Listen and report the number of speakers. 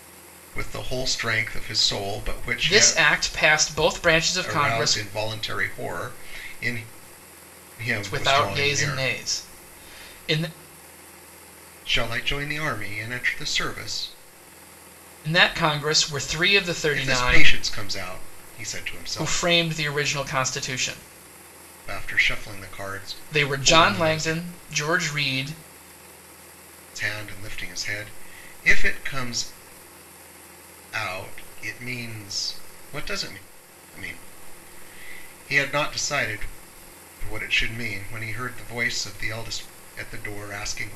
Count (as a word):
two